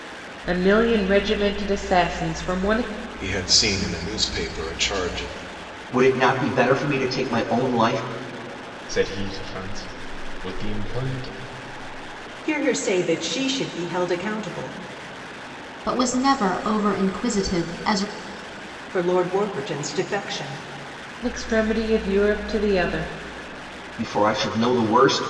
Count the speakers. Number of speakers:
6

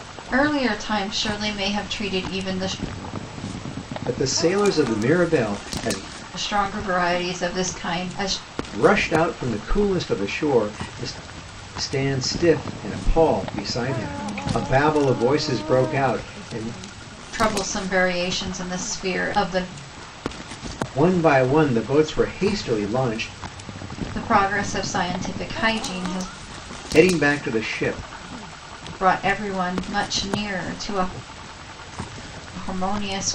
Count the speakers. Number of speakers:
2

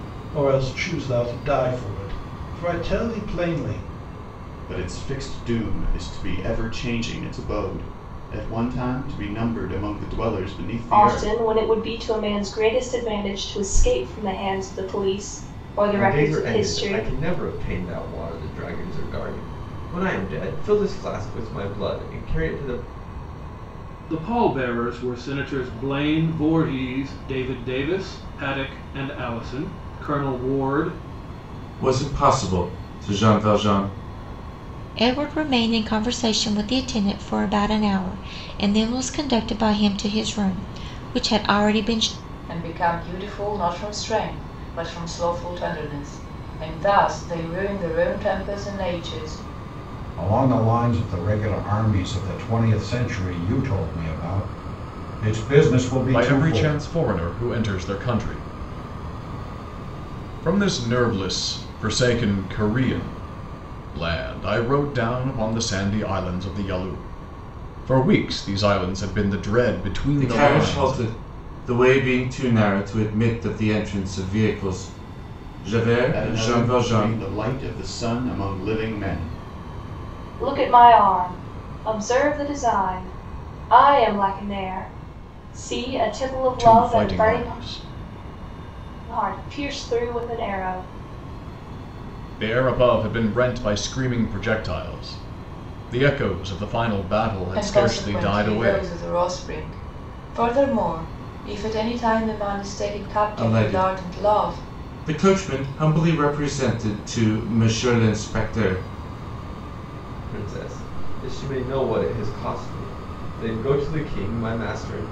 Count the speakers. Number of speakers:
10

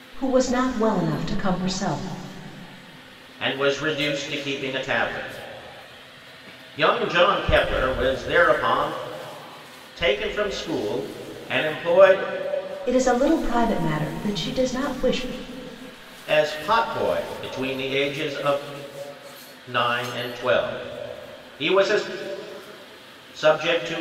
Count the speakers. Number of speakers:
2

